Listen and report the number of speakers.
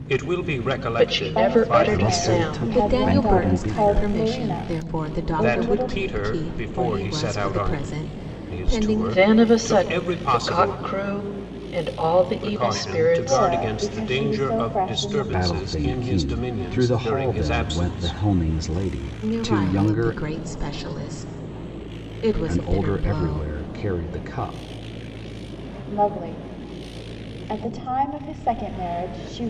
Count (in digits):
5